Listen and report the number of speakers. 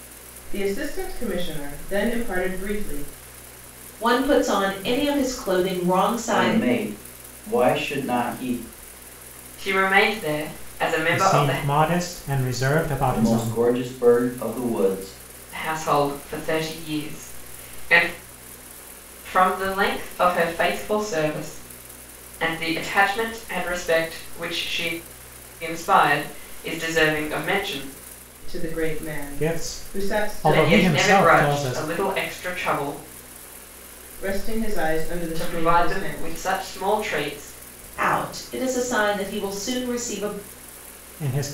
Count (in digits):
5